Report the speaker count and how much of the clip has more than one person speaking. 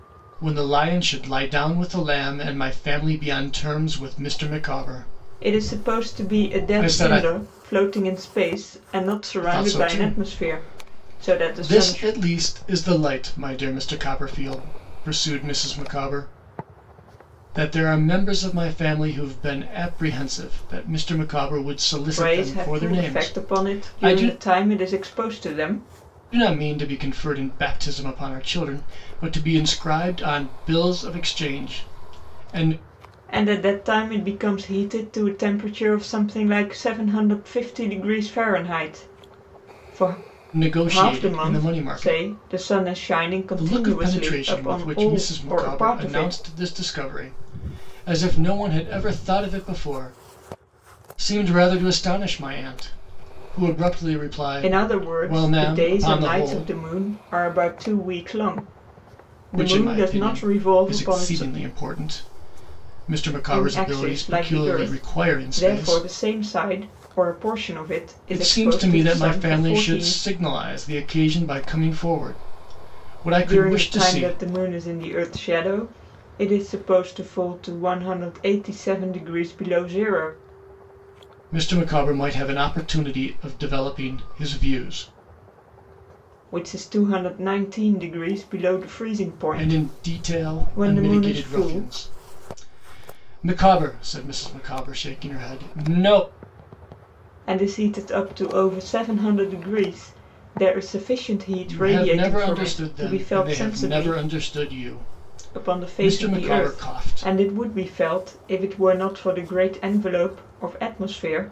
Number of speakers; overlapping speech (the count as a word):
two, about 24%